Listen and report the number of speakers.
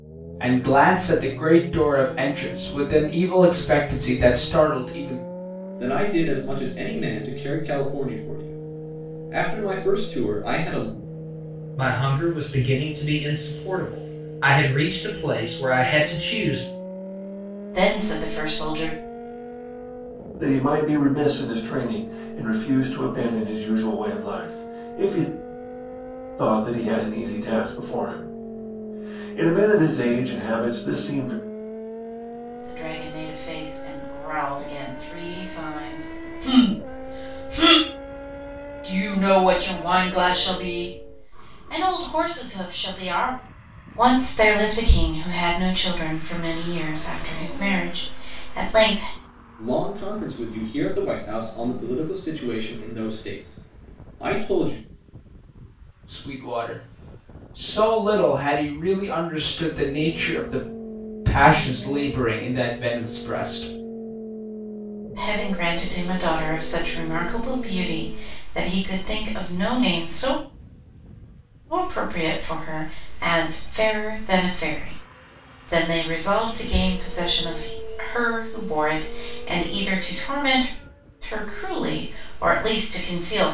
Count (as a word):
five